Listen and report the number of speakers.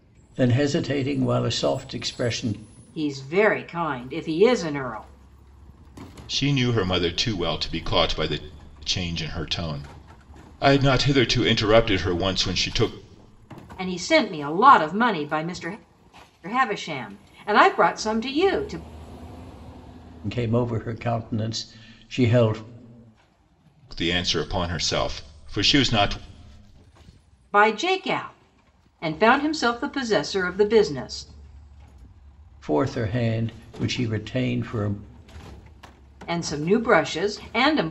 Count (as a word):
three